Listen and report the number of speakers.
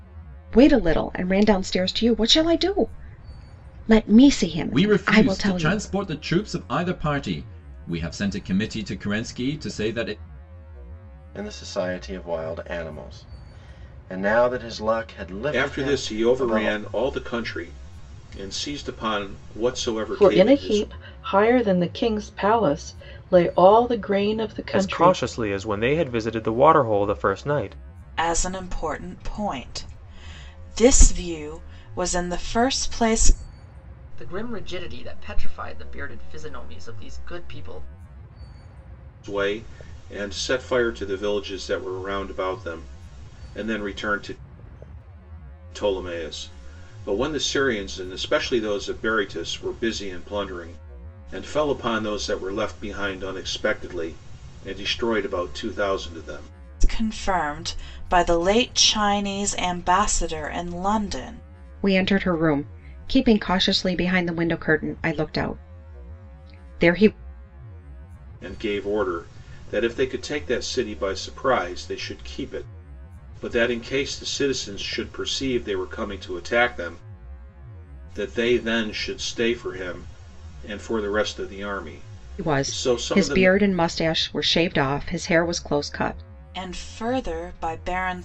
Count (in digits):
8